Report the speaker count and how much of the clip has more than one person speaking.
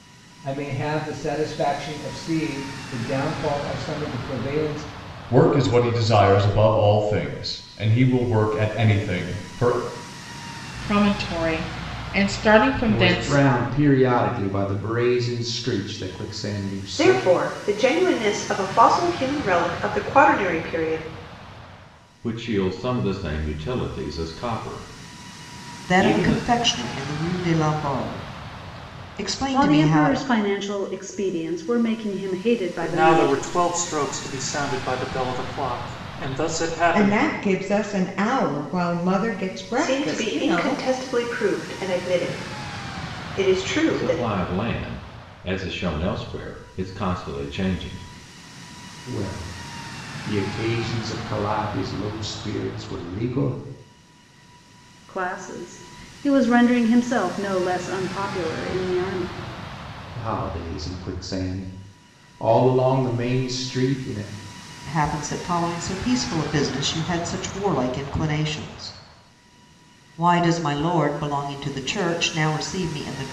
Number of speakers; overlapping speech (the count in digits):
10, about 7%